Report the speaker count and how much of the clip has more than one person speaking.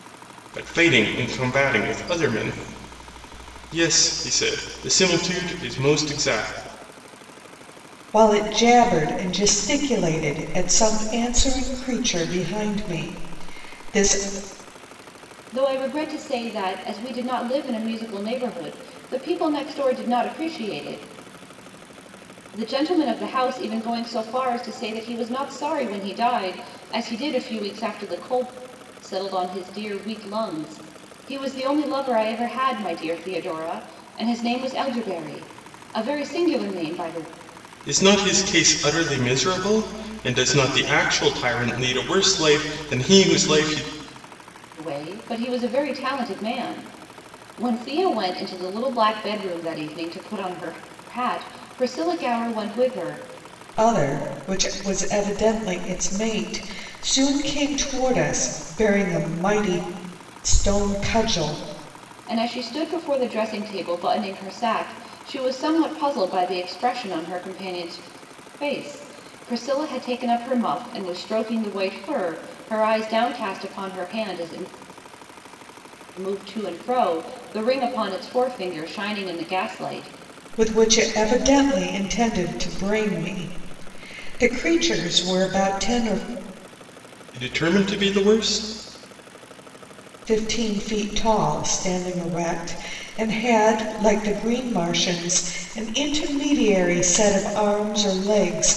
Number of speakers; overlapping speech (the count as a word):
three, no overlap